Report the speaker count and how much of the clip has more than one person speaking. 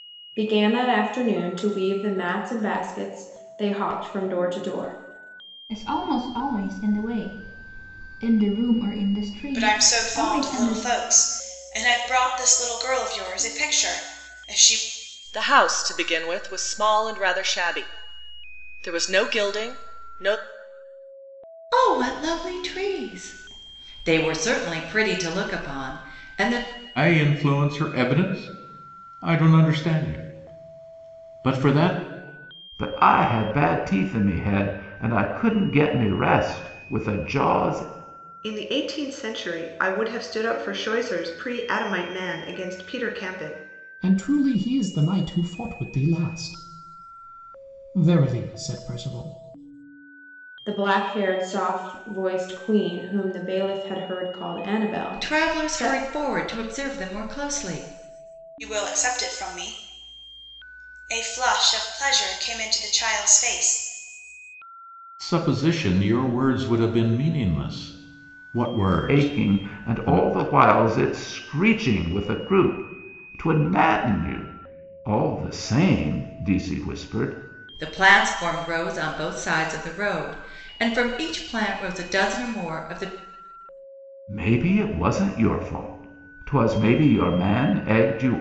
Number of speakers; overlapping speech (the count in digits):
9, about 4%